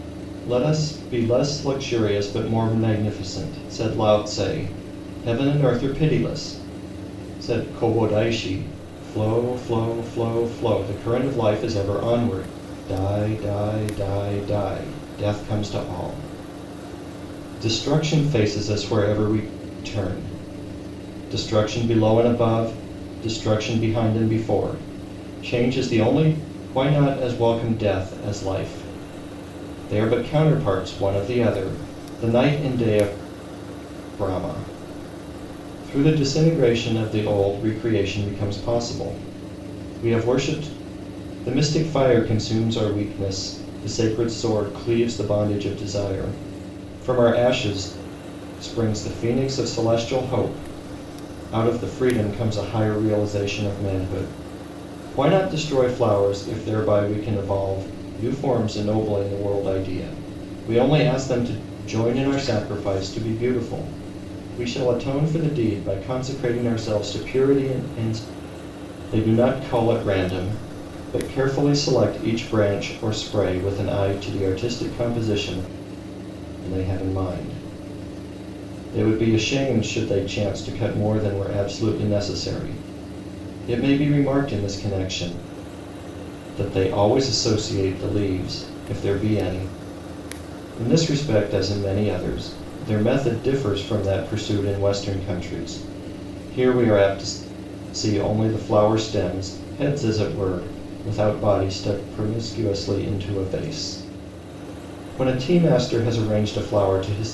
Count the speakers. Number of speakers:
one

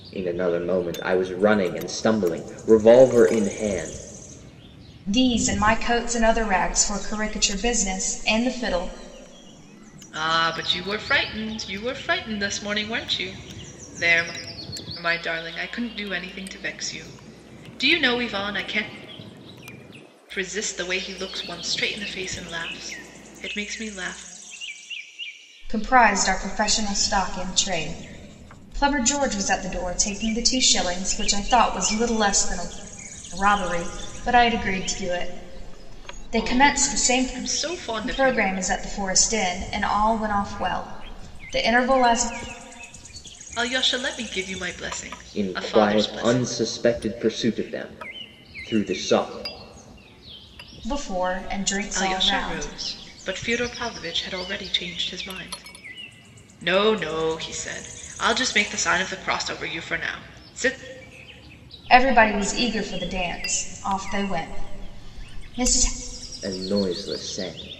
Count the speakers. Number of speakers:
three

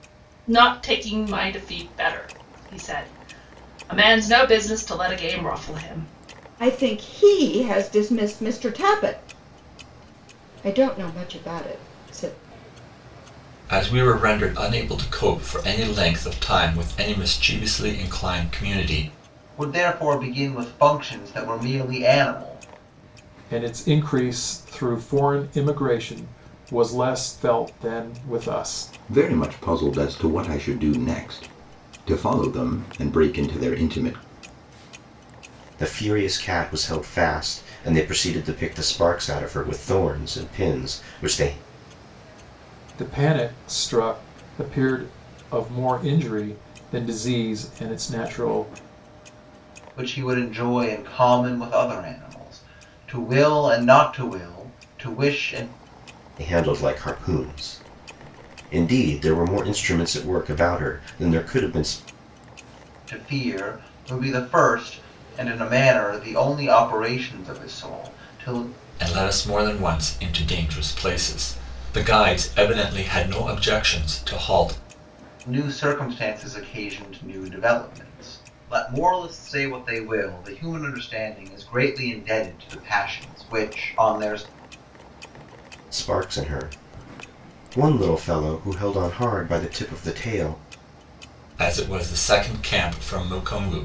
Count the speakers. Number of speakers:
seven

